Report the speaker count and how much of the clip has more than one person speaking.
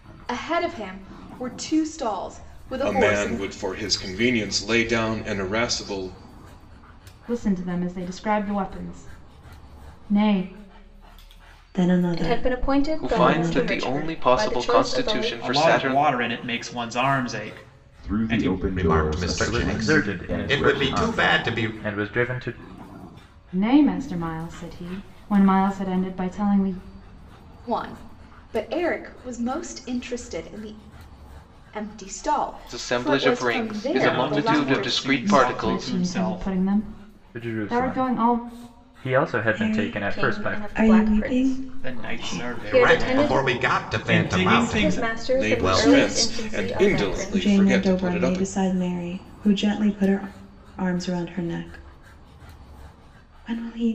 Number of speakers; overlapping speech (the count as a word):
ten, about 41%